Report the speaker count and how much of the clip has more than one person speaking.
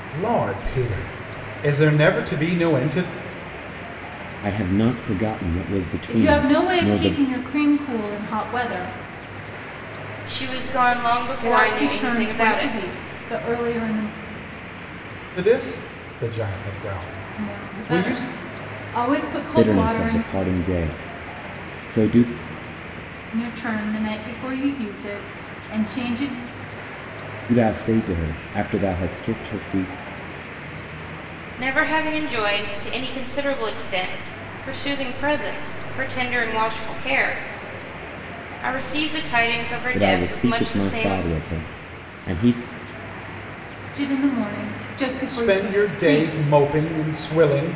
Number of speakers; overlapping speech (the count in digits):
4, about 14%